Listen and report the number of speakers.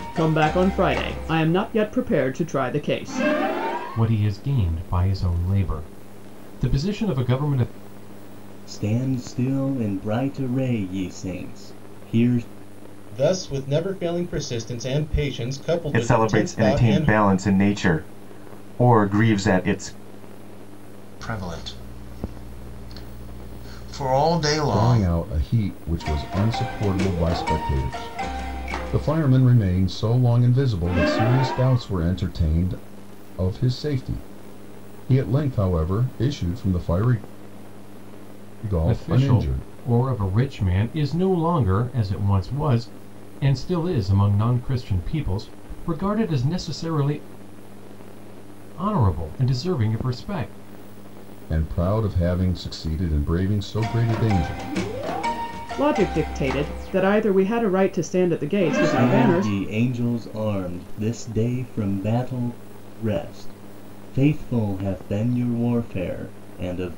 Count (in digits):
7